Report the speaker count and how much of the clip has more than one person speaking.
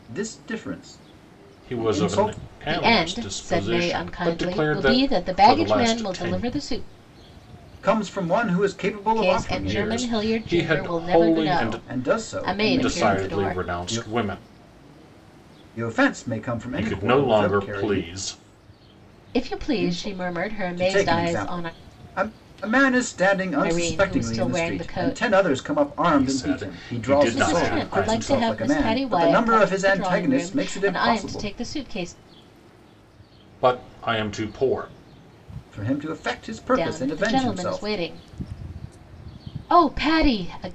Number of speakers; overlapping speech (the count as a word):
three, about 52%